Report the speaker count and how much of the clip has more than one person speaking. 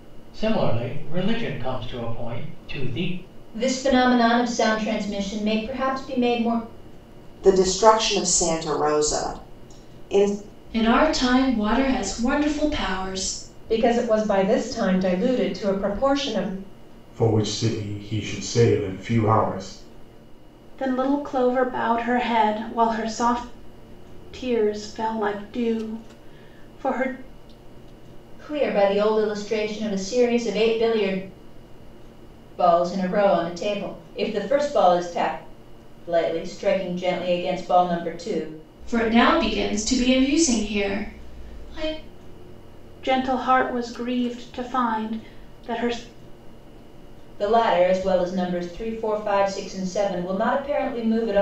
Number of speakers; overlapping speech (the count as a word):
seven, no overlap